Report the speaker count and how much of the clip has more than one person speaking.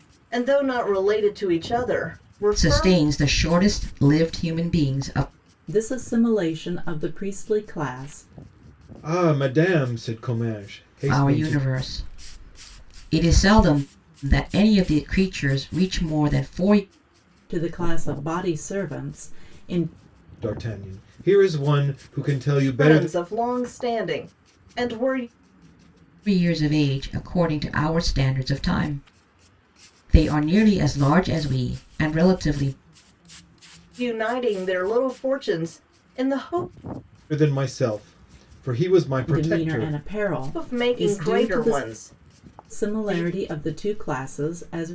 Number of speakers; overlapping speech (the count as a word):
four, about 9%